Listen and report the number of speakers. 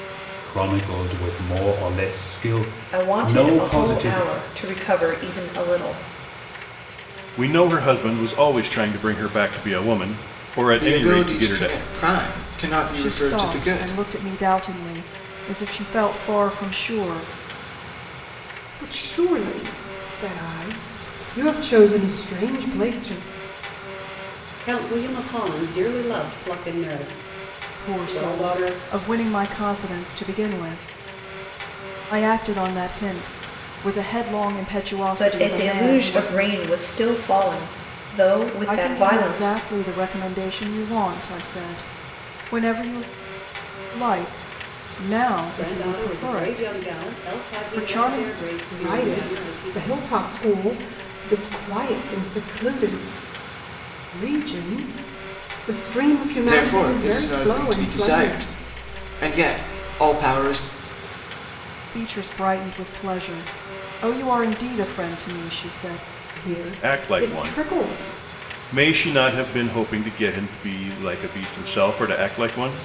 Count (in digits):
7